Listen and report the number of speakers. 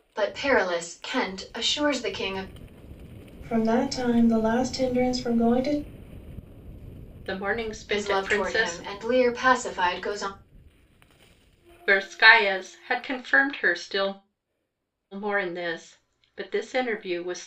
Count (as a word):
three